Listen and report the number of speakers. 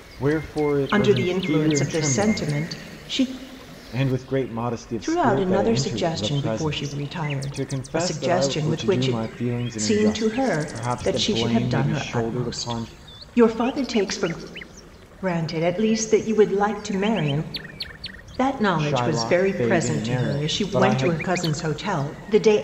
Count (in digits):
2